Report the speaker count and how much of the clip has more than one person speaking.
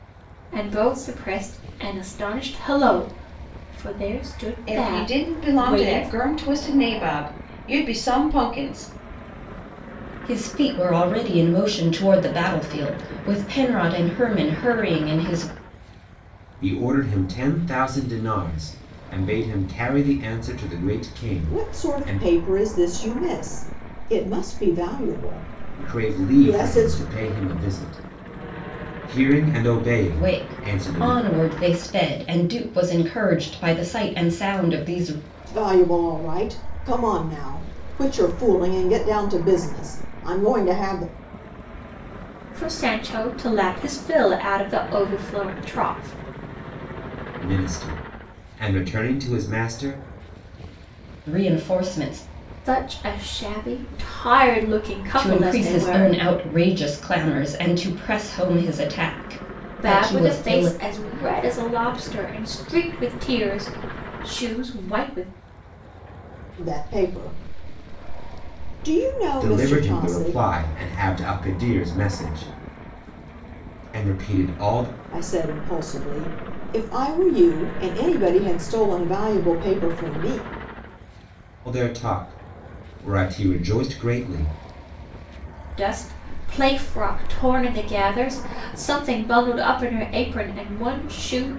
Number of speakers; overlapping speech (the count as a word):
five, about 8%